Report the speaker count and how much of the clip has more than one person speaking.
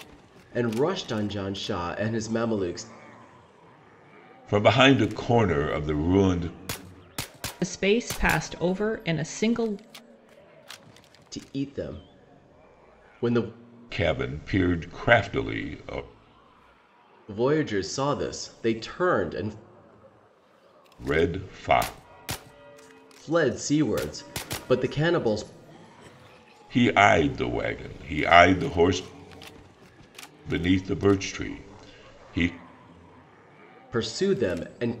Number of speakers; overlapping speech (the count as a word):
three, no overlap